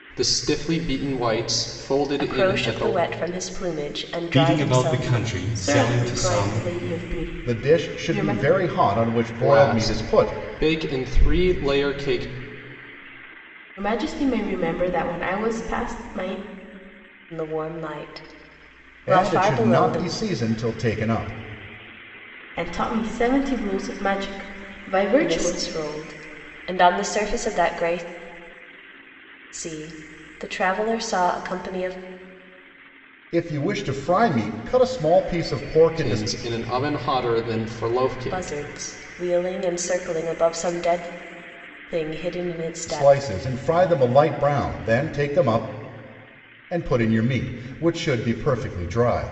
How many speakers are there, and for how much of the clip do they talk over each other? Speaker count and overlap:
five, about 15%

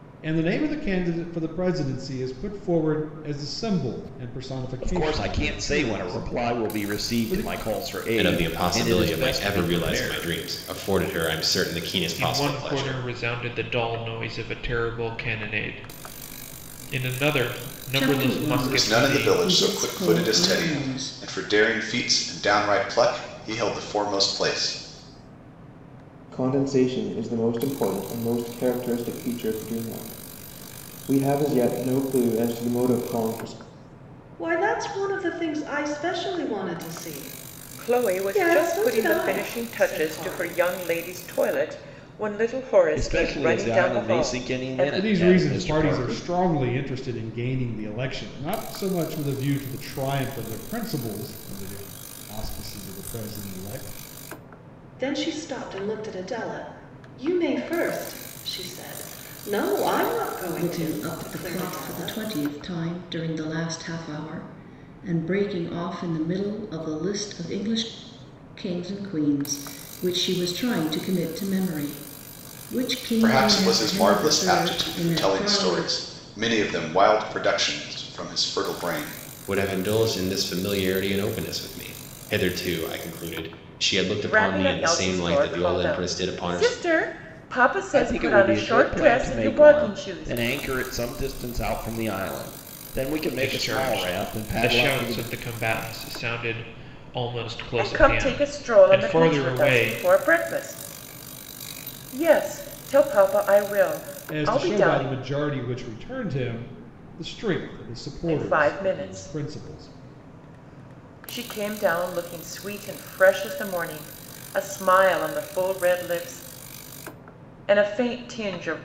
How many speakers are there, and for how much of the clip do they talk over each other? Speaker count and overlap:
nine, about 26%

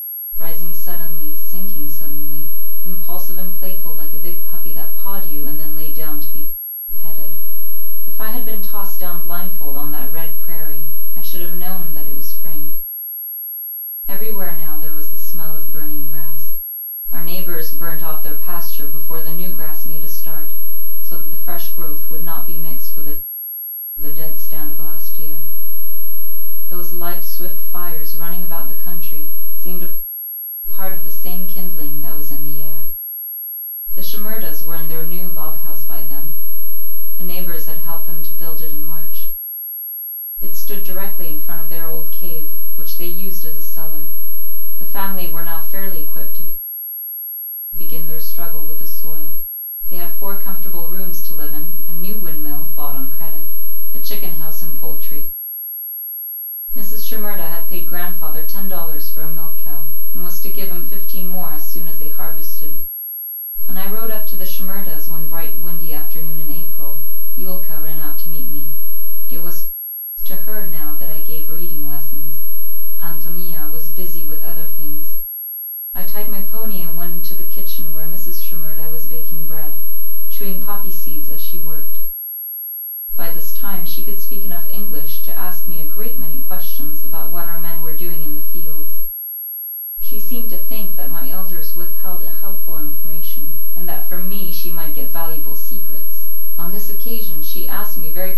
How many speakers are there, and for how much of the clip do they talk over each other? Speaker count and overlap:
one, no overlap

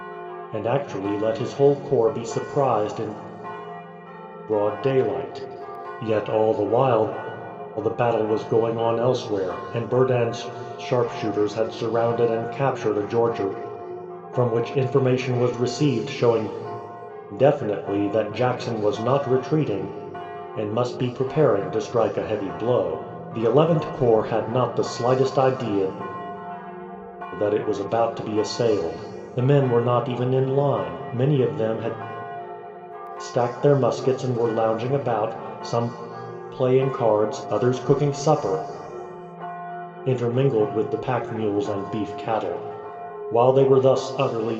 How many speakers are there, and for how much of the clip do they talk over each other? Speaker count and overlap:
one, no overlap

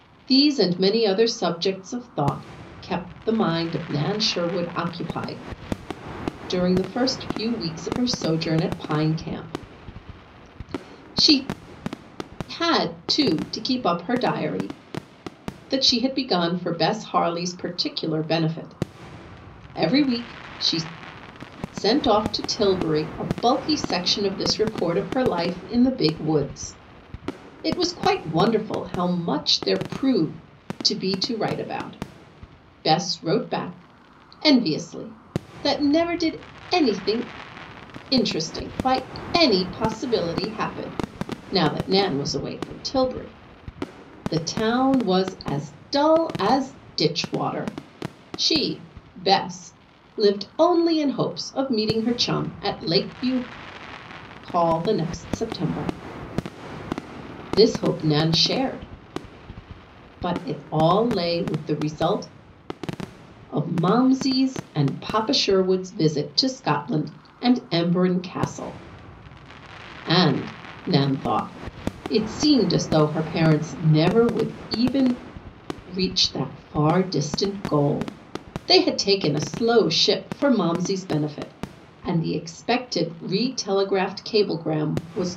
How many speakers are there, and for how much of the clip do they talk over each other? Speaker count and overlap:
one, no overlap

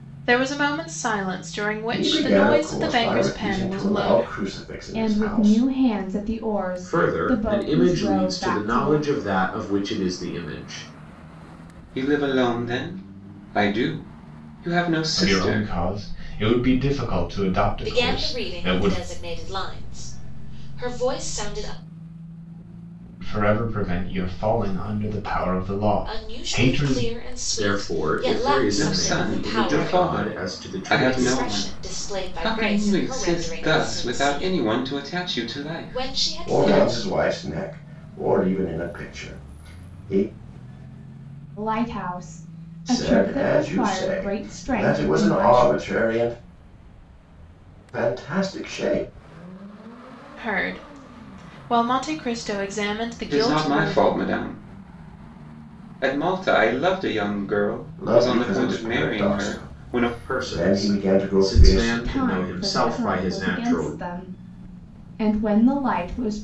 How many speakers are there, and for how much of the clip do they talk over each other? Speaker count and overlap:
seven, about 40%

